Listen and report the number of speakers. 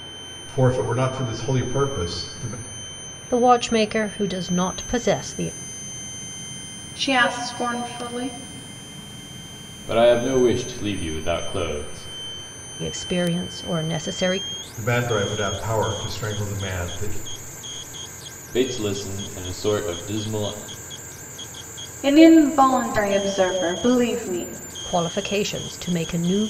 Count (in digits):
4